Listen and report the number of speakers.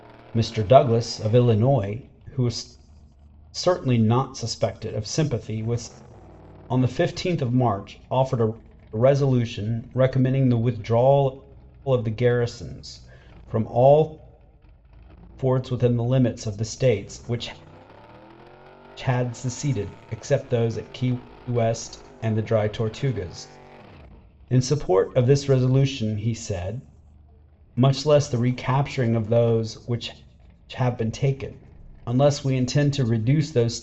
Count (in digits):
1